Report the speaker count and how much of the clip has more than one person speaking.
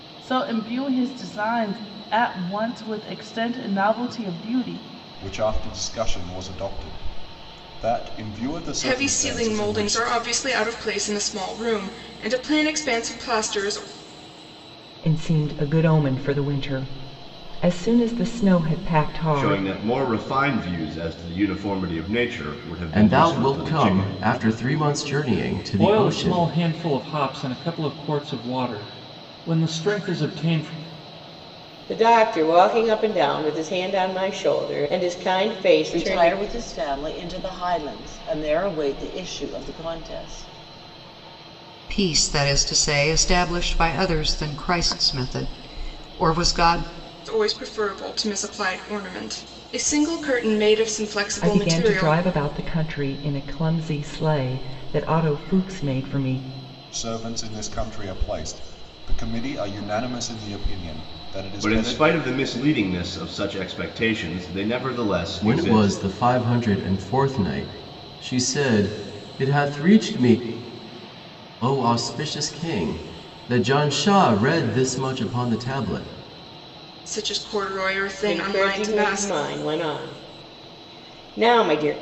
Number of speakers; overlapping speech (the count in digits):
10, about 9%